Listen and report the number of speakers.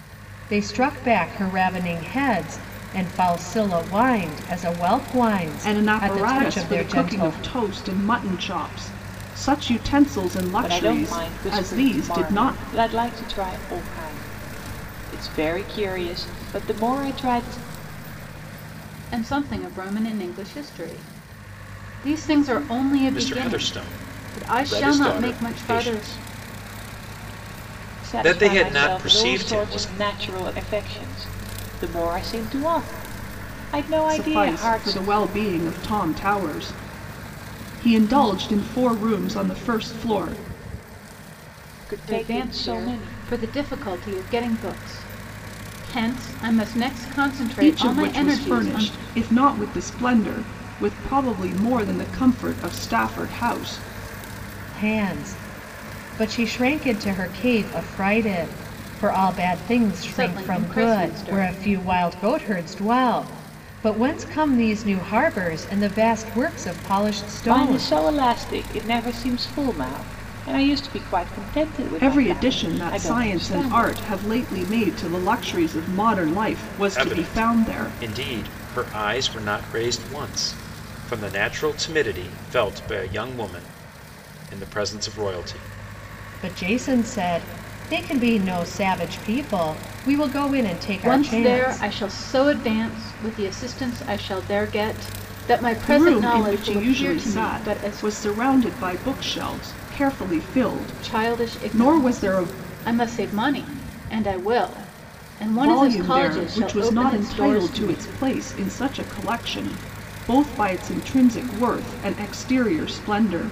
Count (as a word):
five